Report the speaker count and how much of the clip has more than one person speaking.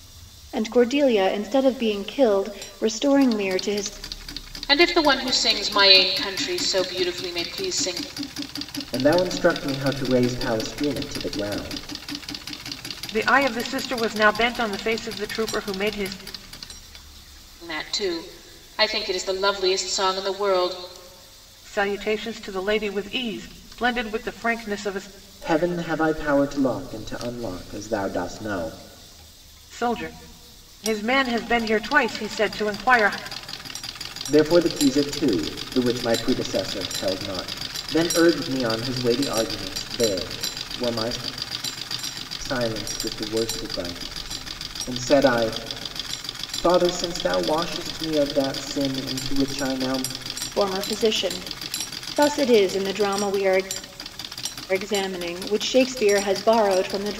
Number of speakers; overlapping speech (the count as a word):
four, no overlap